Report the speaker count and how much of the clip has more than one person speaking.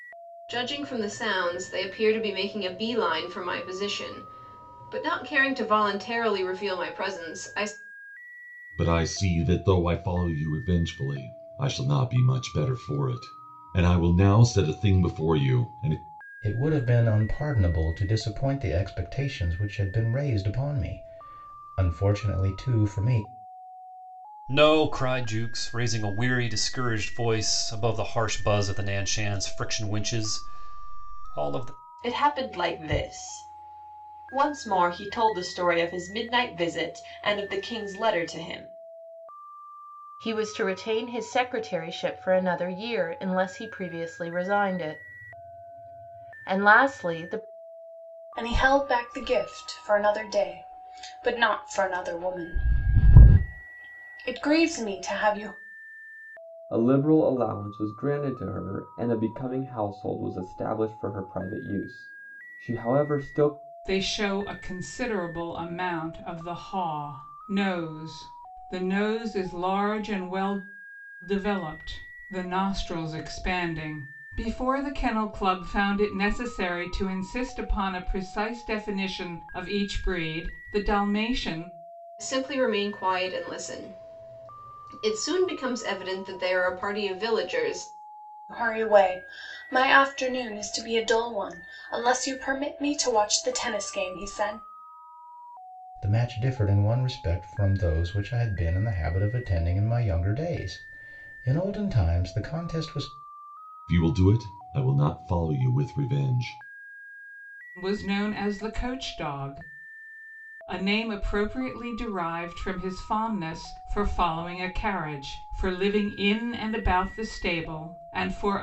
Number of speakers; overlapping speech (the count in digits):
9, no overlap